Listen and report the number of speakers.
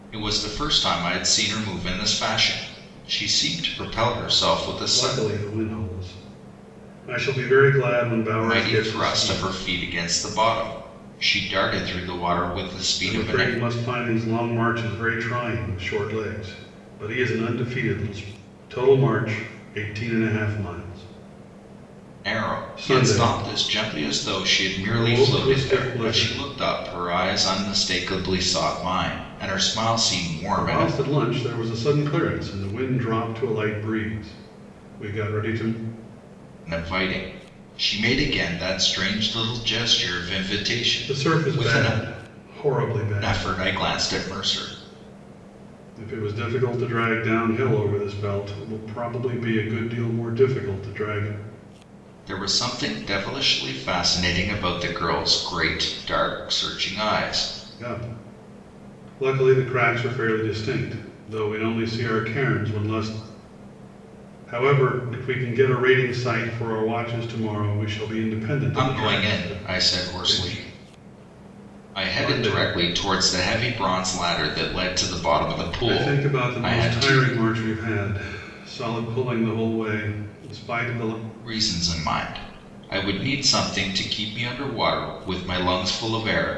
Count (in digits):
2